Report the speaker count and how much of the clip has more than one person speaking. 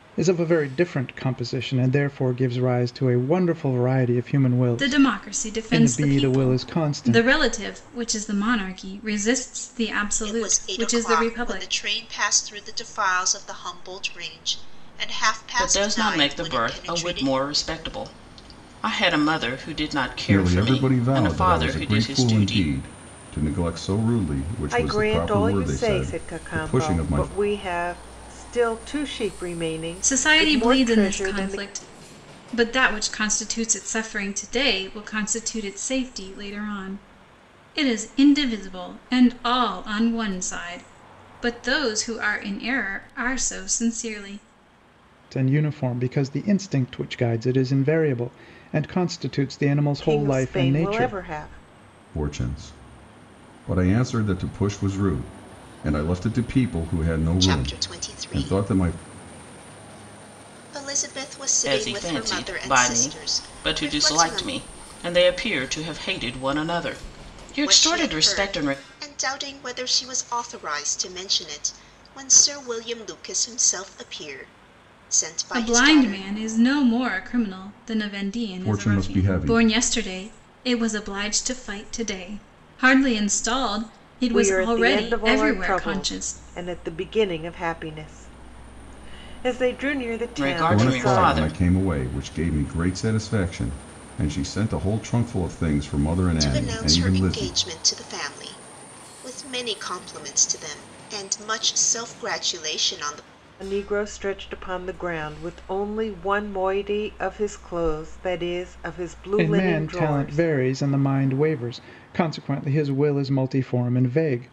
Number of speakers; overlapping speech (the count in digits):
6, about 24%